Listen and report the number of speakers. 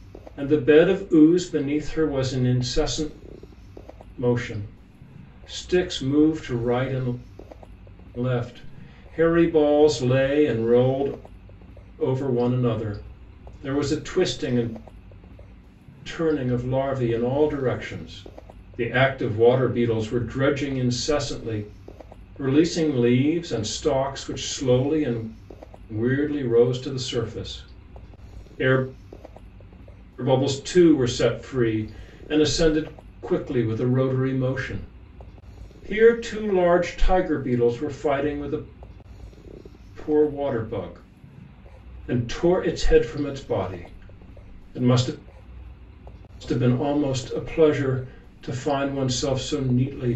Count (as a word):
one